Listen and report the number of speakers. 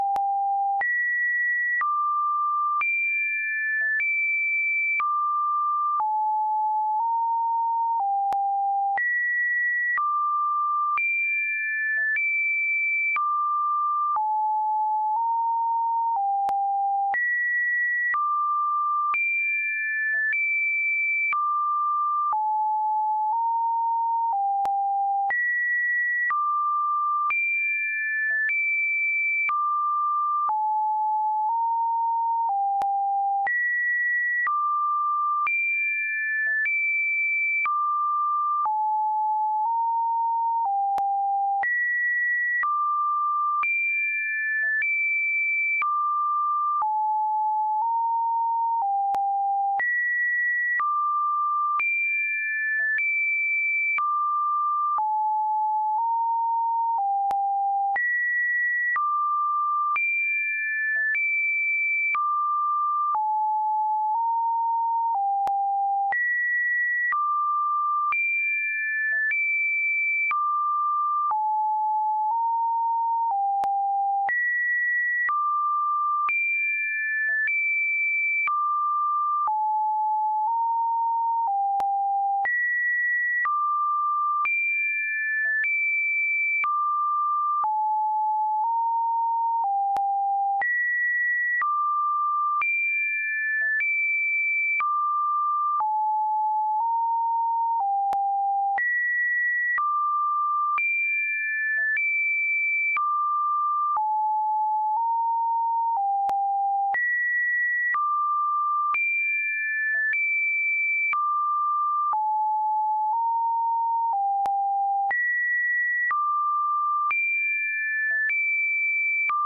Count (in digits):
0